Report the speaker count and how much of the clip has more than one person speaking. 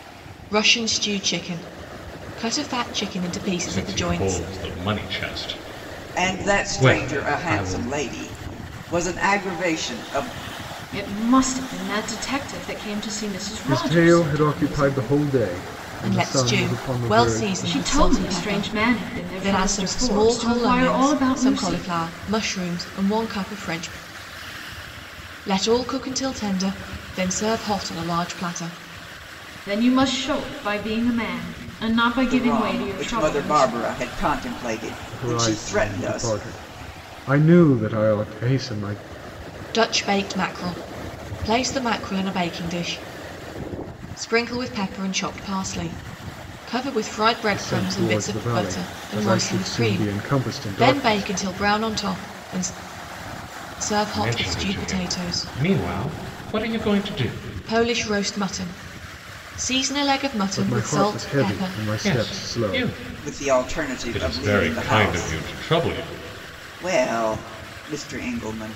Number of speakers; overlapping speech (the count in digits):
5, about 33%